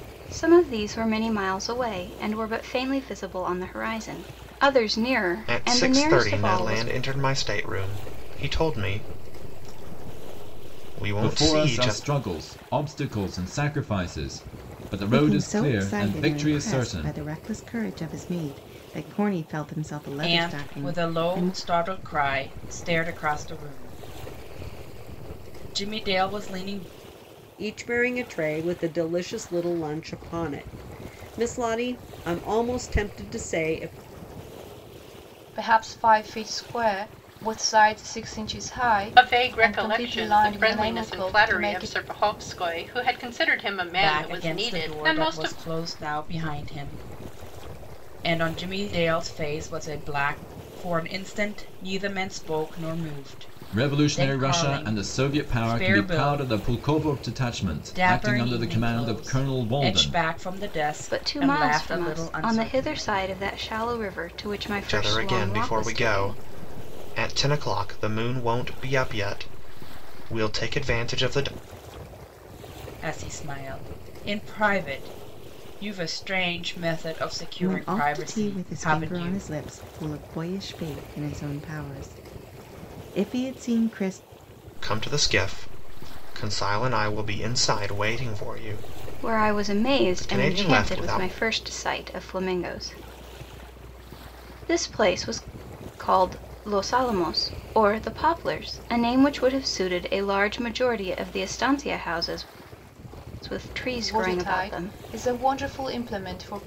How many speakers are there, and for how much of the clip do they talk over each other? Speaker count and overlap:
eight, about 22%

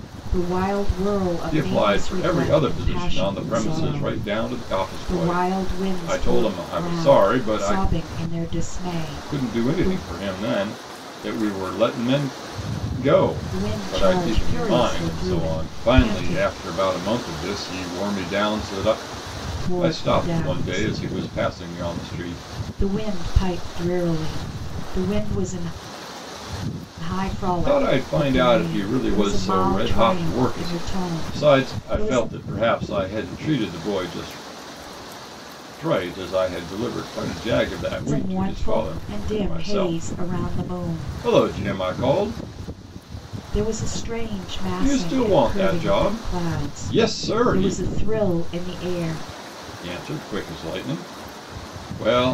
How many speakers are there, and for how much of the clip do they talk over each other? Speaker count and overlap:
two, about 40%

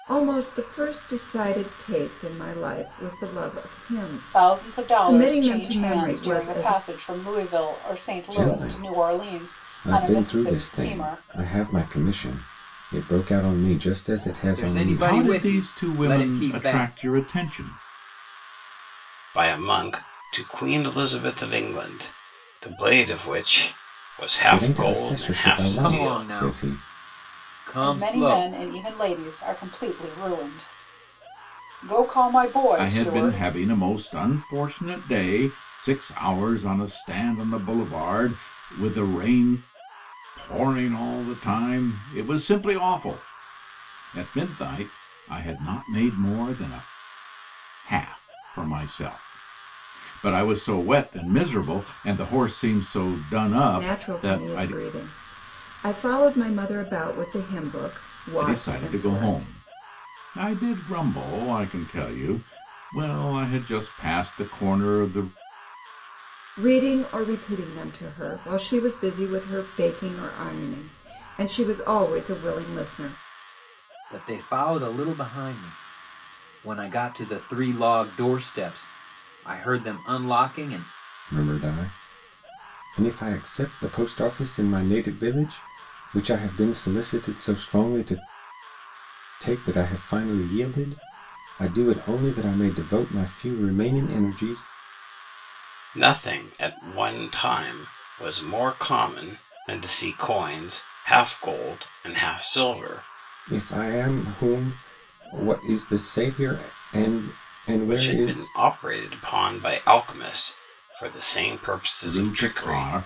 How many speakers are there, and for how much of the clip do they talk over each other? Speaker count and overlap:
six, about 14%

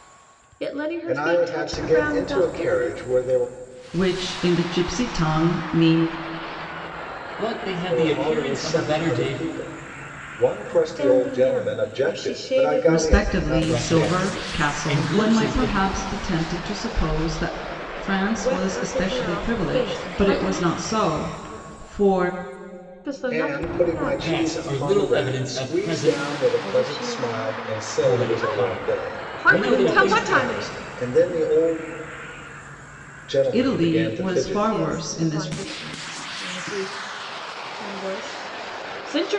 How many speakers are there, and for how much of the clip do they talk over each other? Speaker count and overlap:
four, about 51%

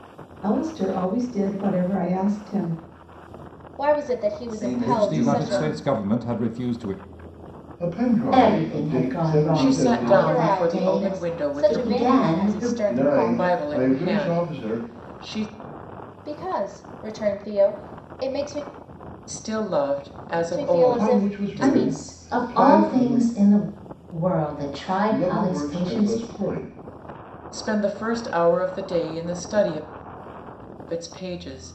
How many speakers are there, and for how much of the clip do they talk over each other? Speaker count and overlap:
seven, about 37%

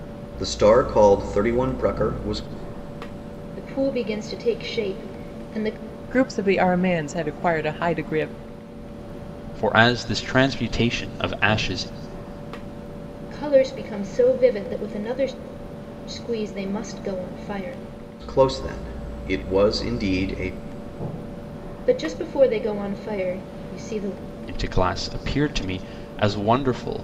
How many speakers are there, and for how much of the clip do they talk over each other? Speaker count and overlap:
four, no overlap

